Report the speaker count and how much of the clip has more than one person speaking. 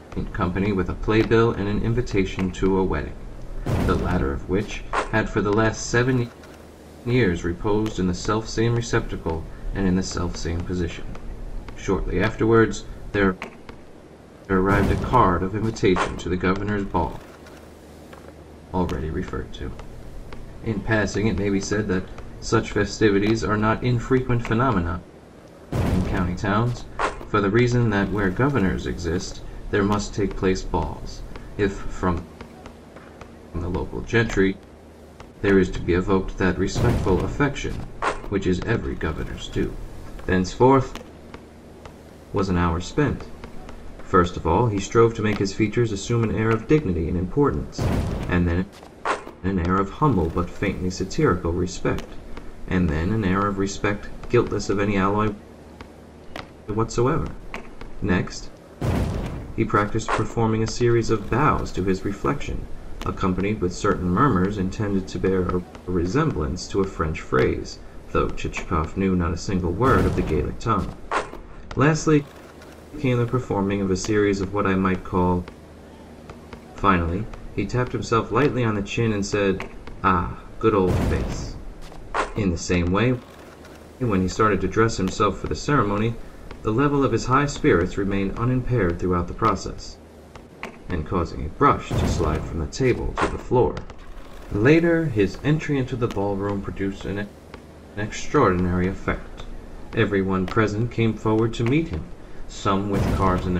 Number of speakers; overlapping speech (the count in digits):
1, no overlap